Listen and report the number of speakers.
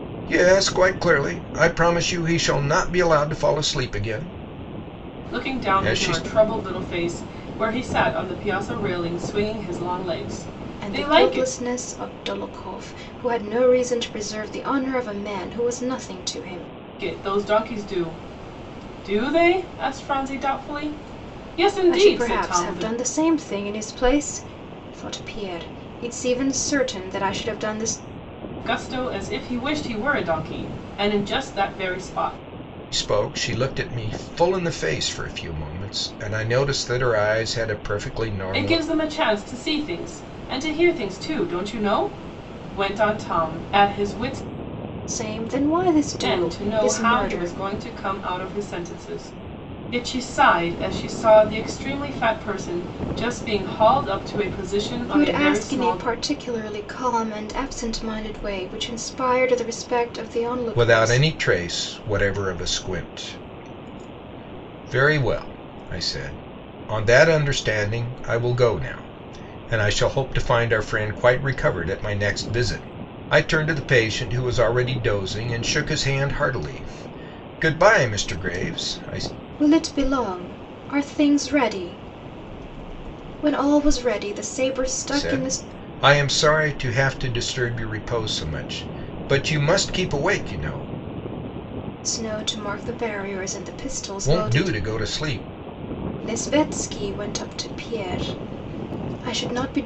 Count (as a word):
three